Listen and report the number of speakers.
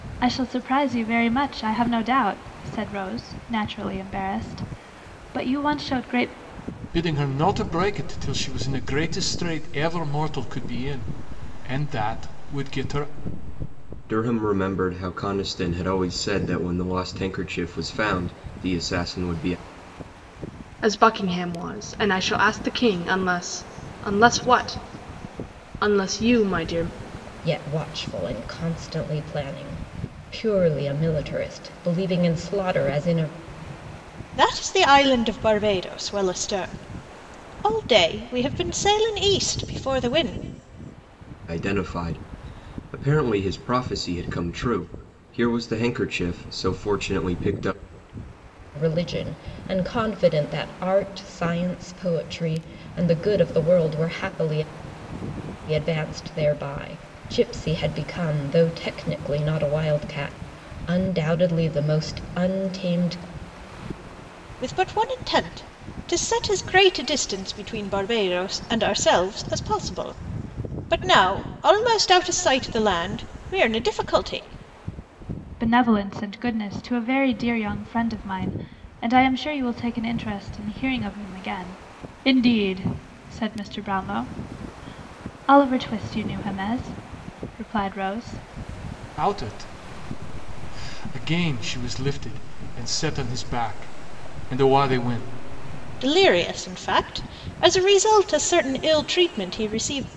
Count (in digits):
6